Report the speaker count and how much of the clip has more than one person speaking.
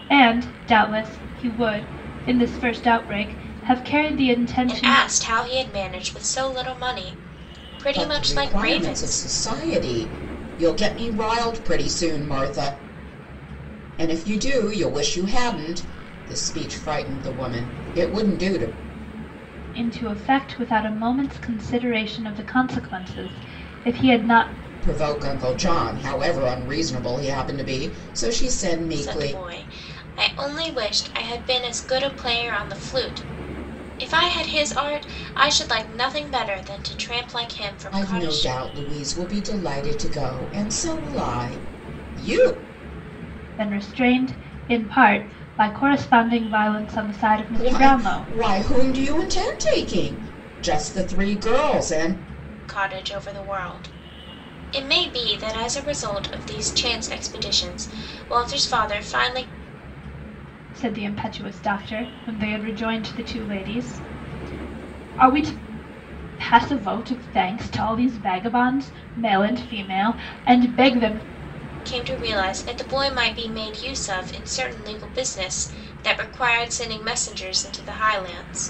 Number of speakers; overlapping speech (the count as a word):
three, about 4%